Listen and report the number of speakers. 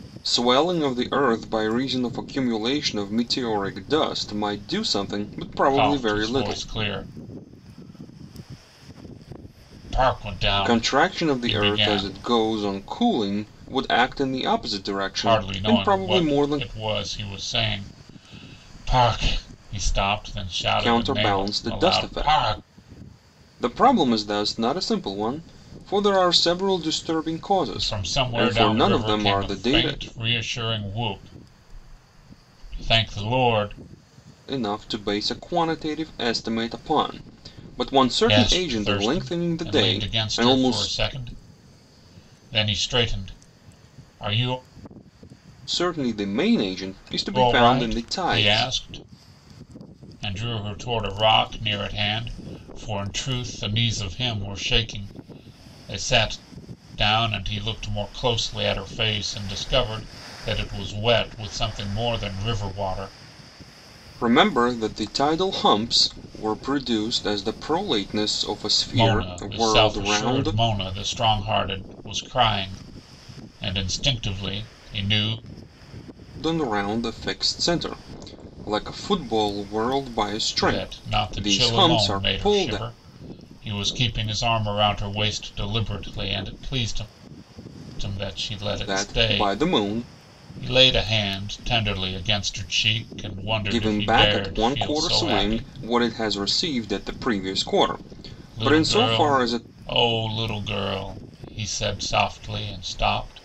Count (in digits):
2